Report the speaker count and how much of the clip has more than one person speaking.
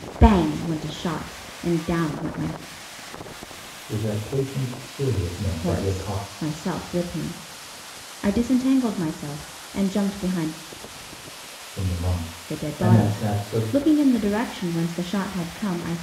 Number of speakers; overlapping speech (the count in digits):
2, about 12%